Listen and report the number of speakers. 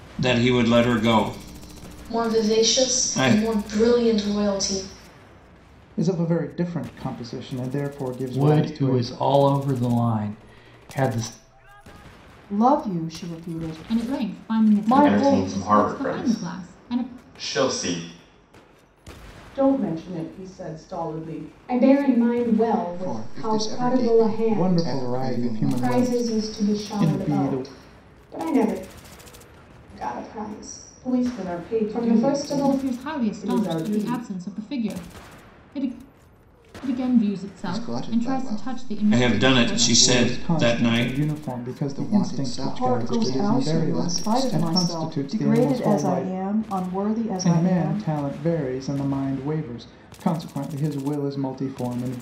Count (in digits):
10